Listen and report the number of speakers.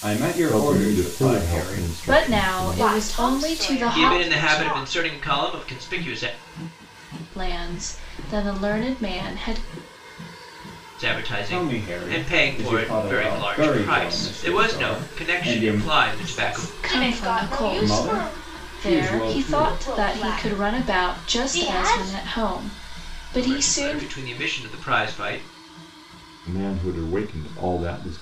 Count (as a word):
five